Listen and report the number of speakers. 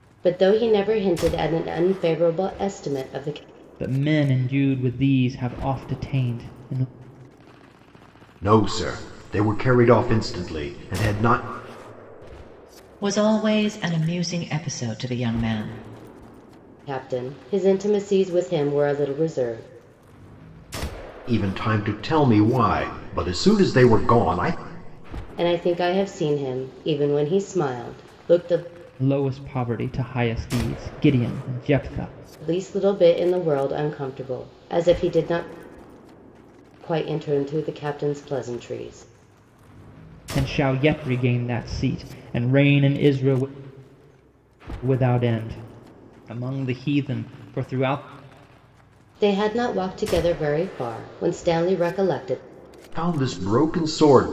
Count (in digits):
4